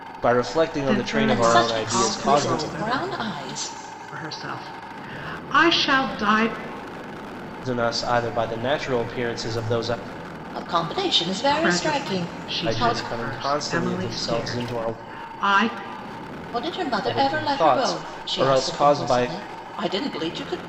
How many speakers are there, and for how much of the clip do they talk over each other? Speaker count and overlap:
3, about 39%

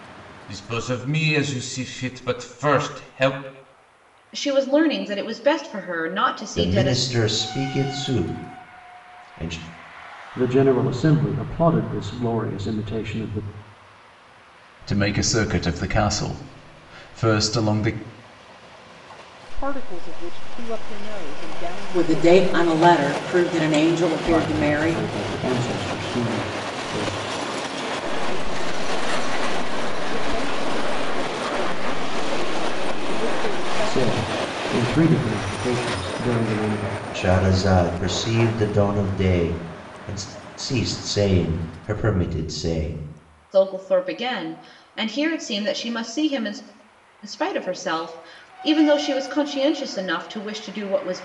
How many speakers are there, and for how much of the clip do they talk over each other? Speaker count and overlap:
7, about 5%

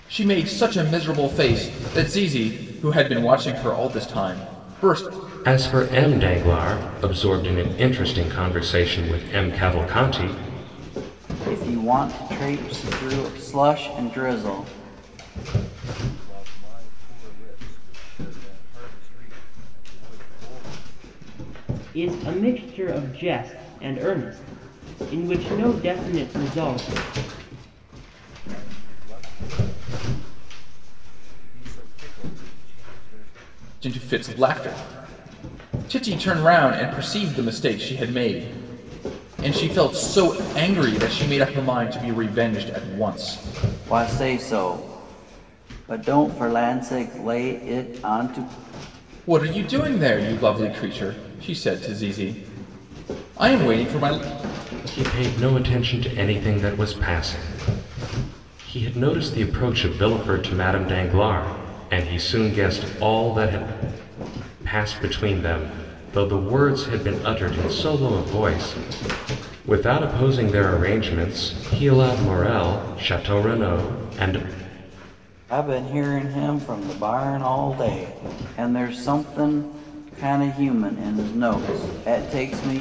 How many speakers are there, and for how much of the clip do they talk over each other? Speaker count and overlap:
5, no overlap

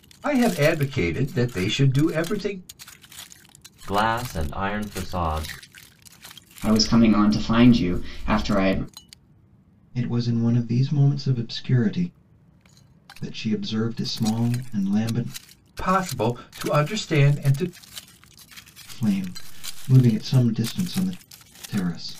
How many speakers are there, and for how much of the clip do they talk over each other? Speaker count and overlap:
4, no overlap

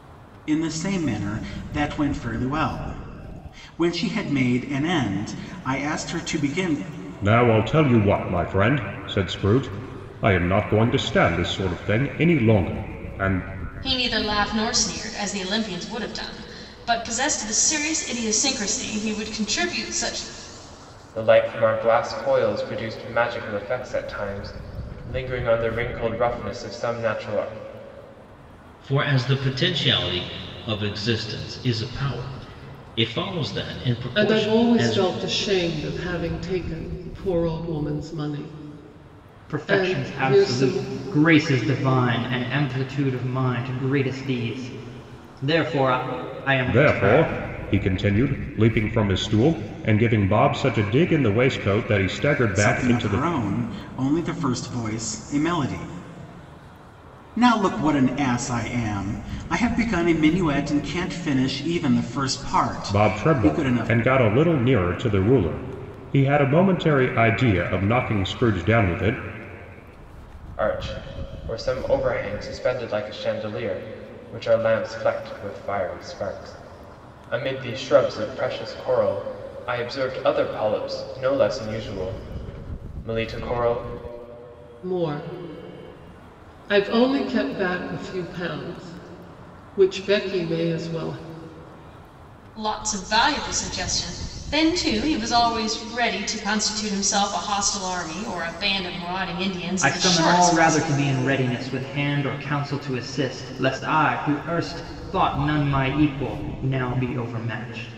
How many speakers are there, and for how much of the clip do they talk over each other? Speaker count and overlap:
7, about 6%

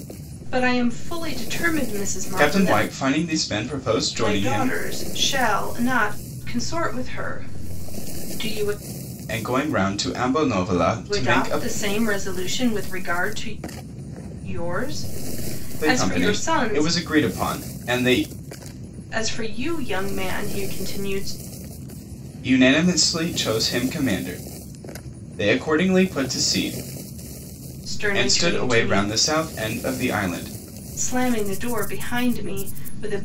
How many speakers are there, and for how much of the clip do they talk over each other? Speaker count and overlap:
2, about 12%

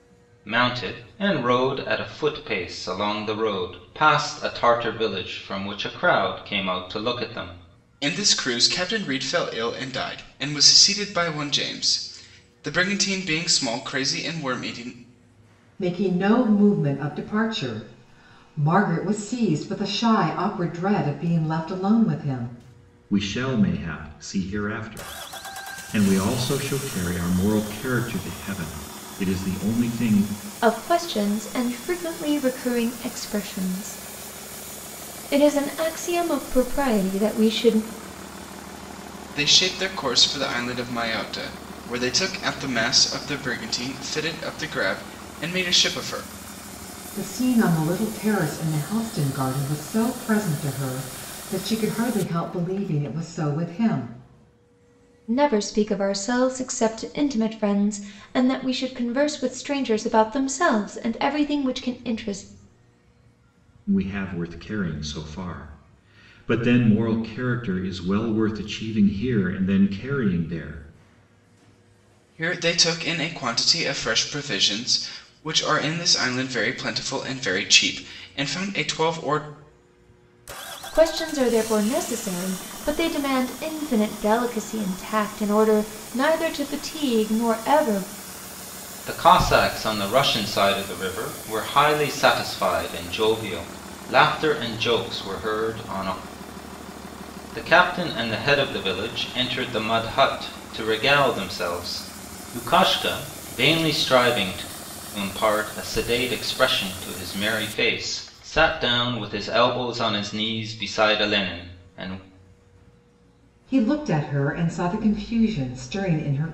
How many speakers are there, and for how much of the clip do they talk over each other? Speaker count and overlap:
5, no overlap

